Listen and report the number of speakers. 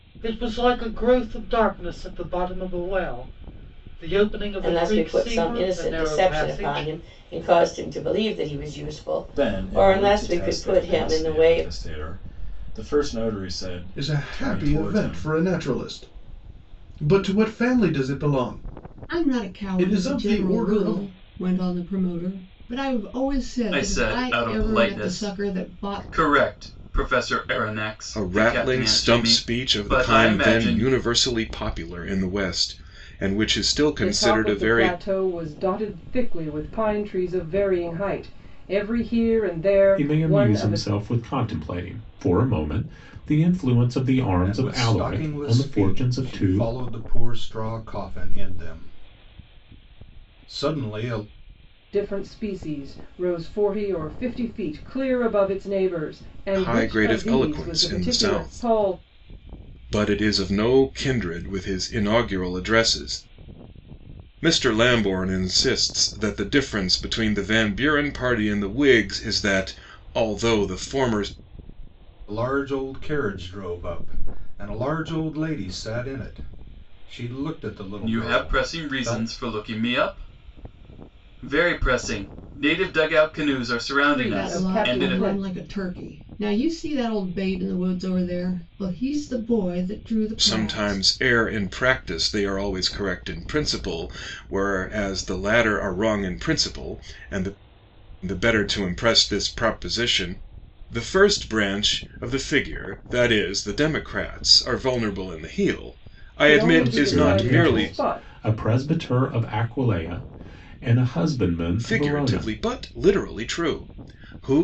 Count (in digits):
10